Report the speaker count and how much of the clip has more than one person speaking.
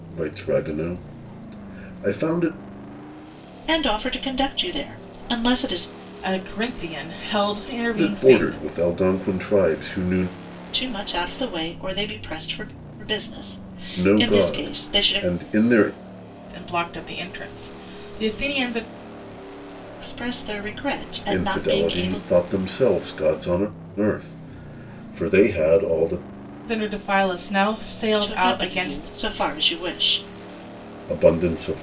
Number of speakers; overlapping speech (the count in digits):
3, about 12%